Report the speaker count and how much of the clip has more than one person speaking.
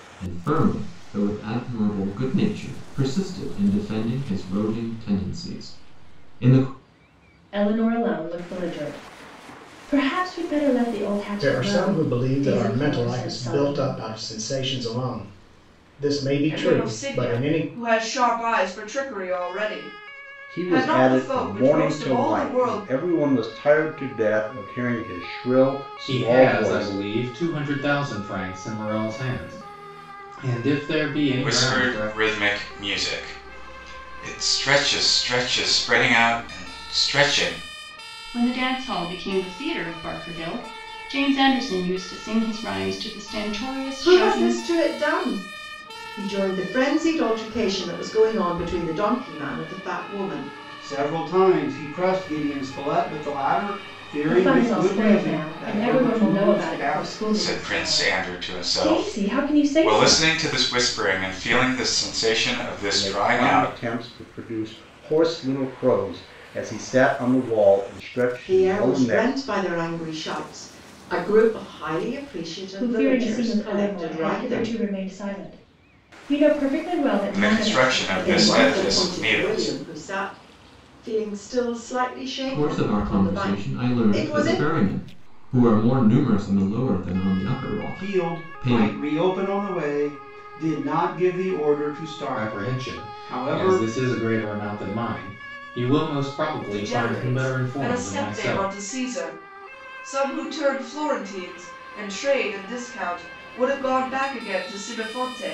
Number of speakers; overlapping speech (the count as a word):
ten, about 26%